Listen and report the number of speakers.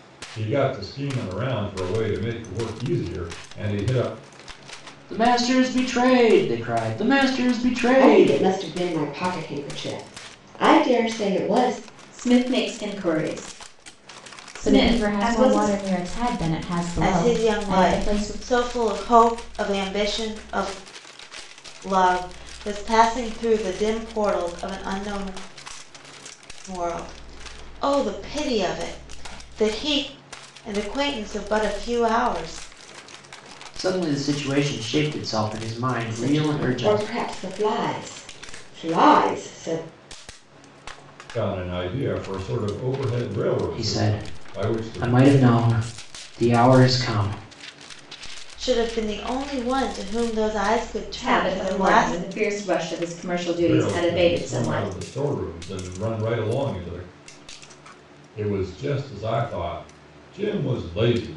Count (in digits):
6